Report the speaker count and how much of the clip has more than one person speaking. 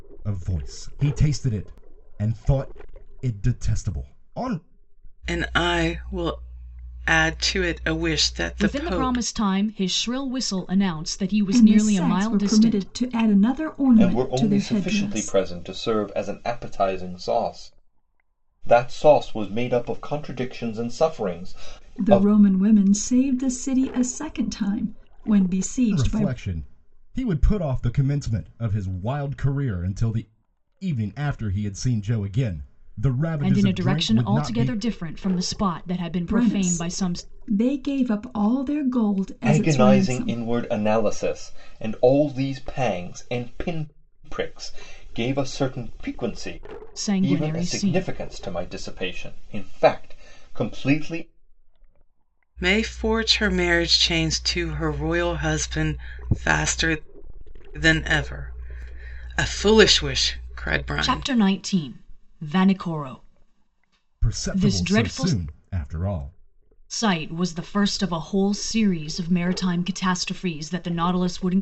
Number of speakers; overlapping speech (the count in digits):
5, about 14%